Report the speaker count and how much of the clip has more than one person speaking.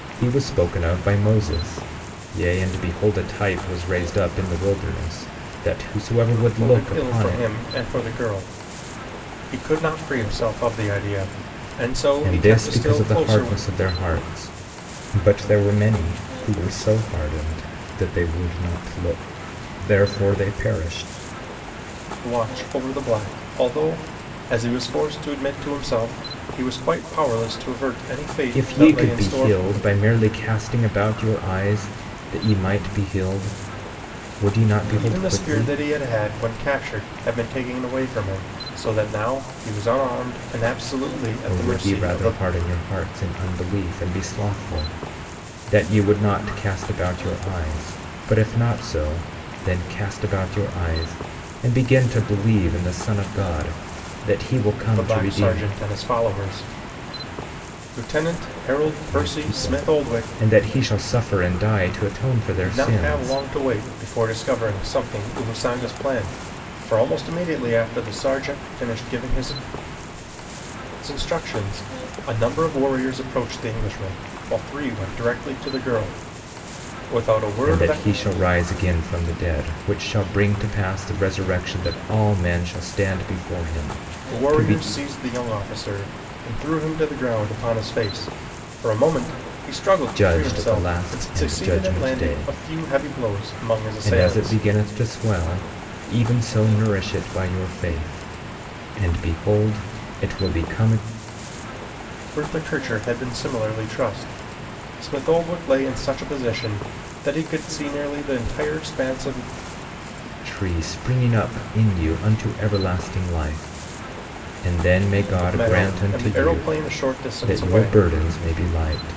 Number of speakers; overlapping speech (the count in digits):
2, about 12%